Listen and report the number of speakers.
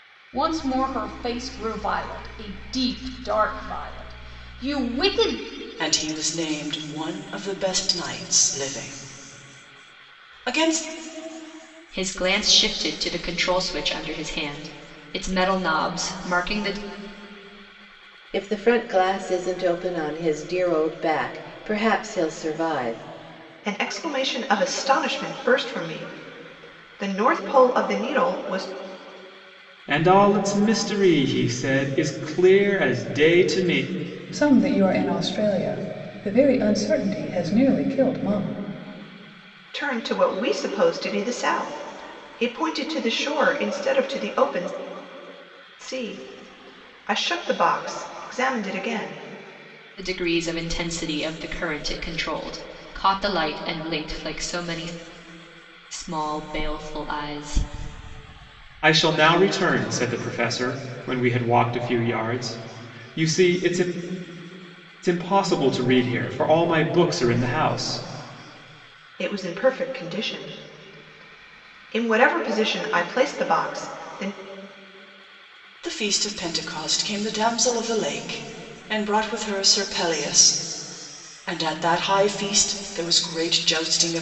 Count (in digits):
7